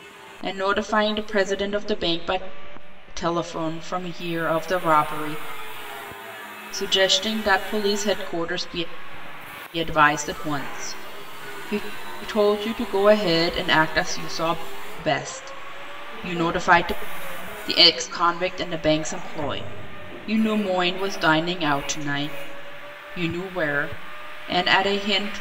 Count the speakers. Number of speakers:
one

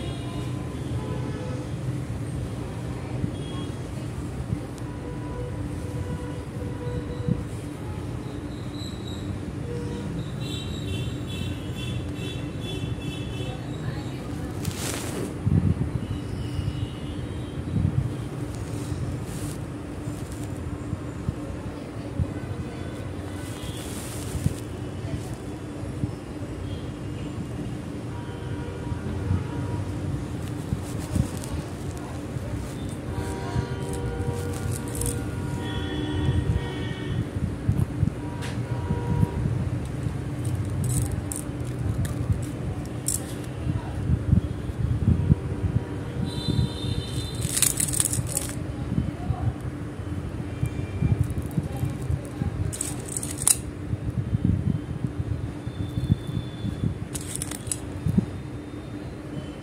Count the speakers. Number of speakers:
zero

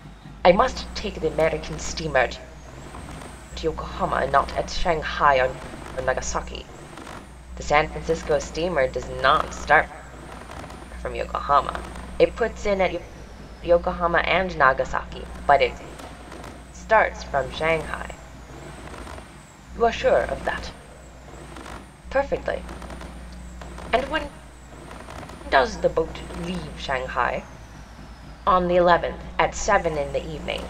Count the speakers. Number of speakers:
one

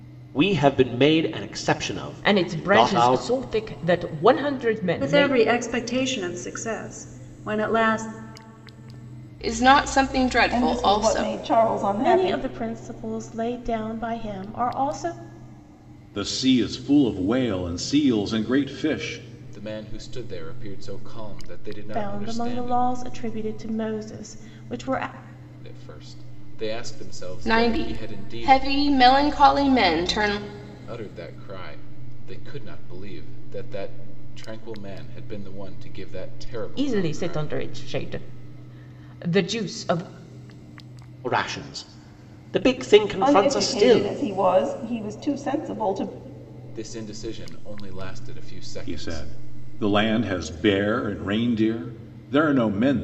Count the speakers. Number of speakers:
eight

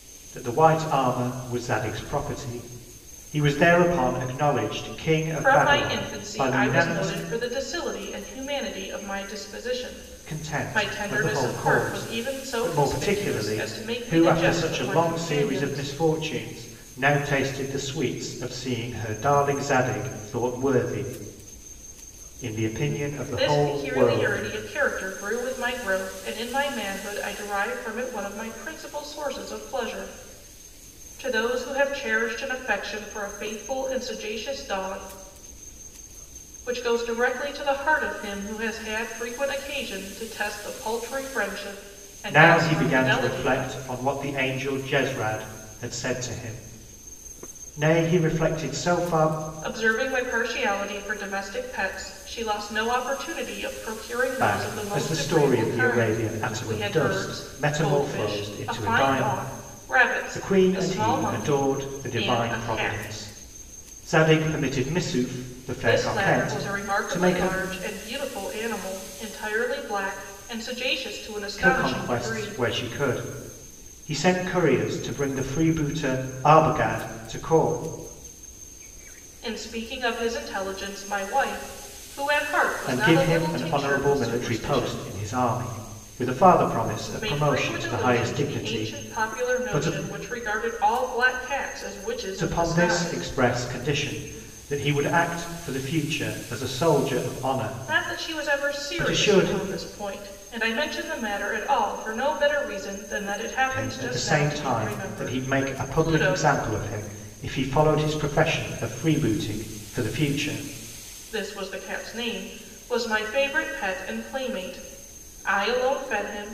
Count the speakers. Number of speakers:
two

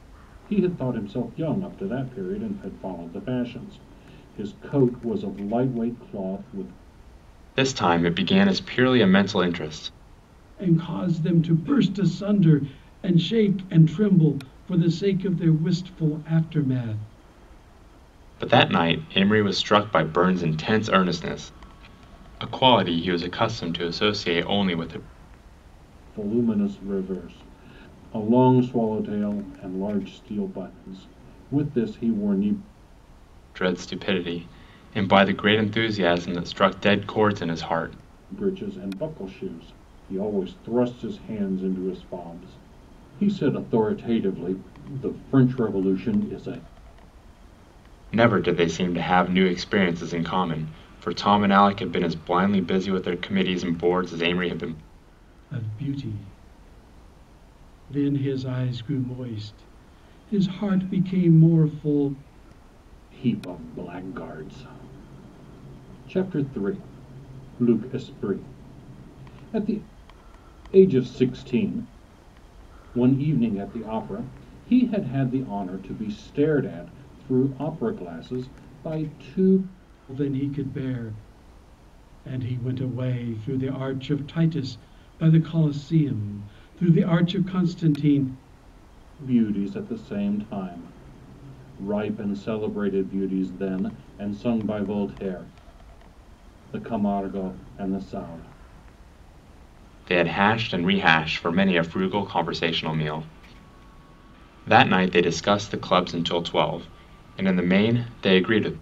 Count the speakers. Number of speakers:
three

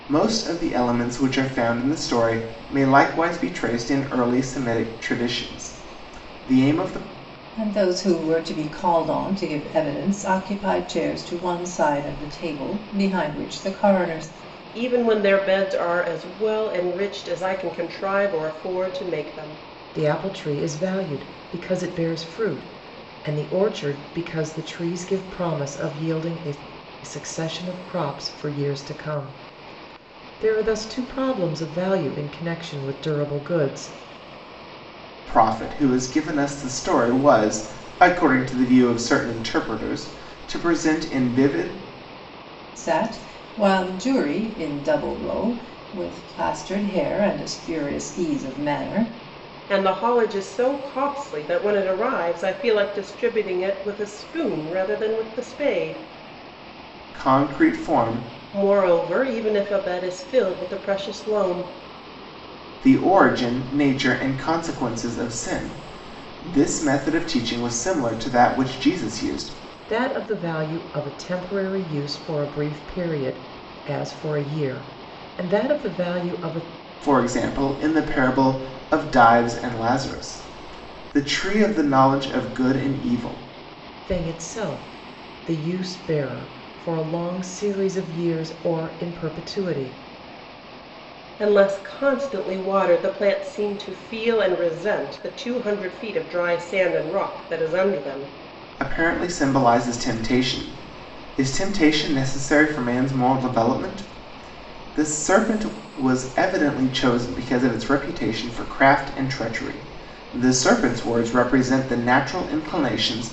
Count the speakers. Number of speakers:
four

